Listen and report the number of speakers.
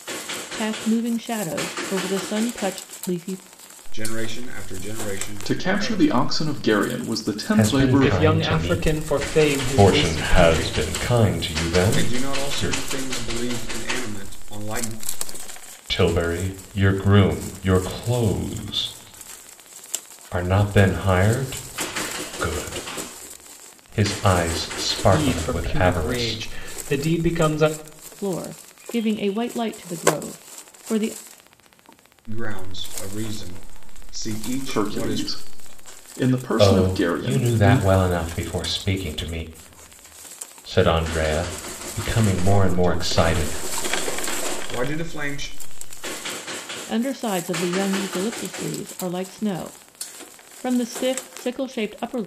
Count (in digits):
5